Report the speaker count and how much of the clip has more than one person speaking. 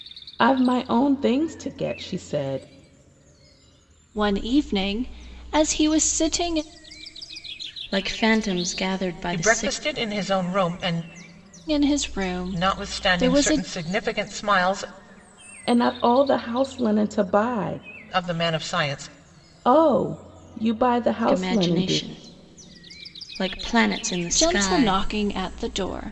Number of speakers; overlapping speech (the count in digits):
4, about 12%